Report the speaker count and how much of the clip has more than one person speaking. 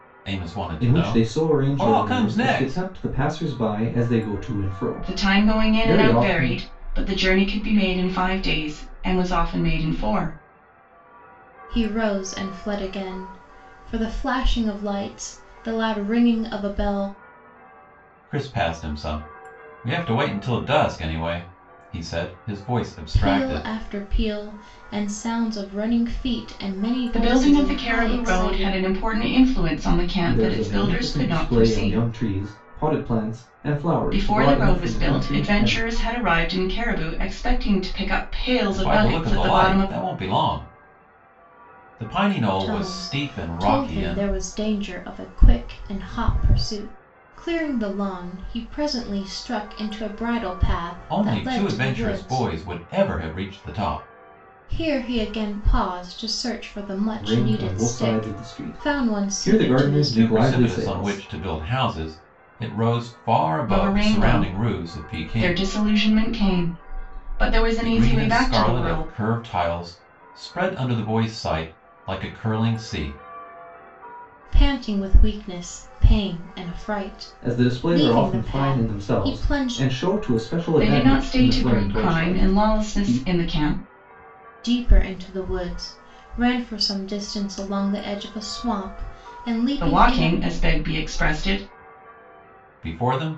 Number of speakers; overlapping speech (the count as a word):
four, about 29%